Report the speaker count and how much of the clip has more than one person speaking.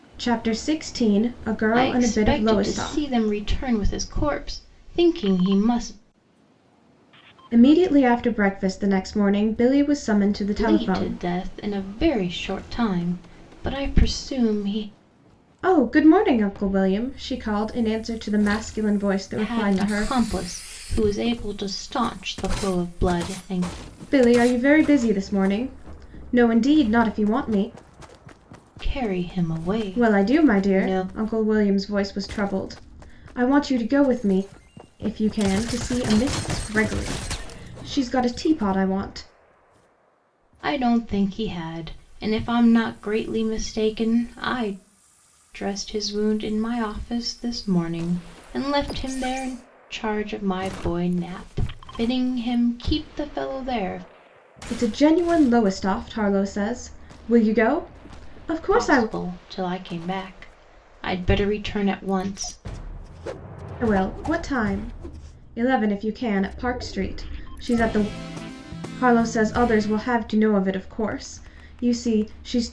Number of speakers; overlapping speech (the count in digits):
2, about 6%